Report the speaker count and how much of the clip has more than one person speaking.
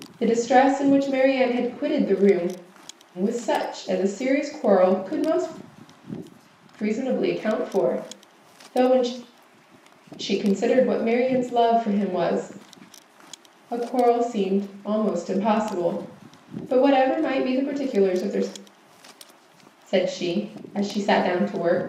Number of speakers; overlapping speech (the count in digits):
1, no overlap